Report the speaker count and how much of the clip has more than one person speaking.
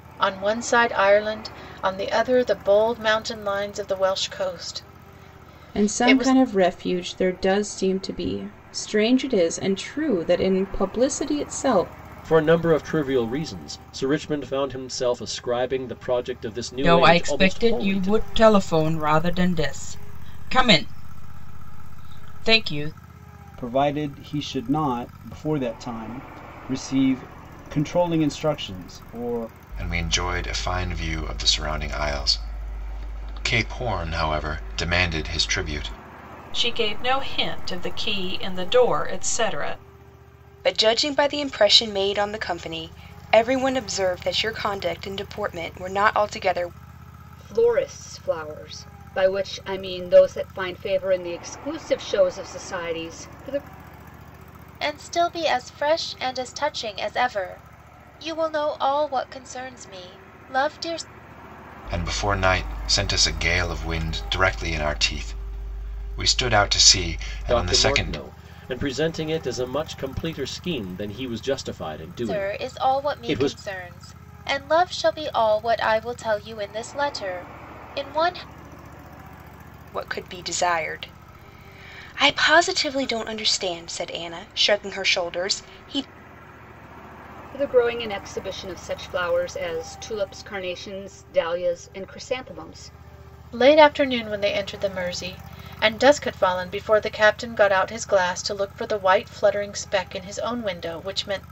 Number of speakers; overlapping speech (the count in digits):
10, about 4%